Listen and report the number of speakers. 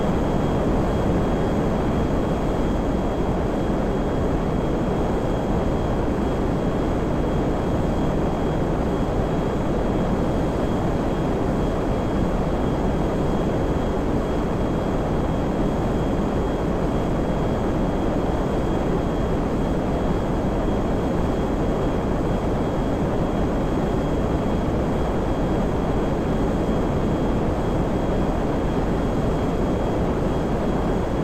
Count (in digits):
0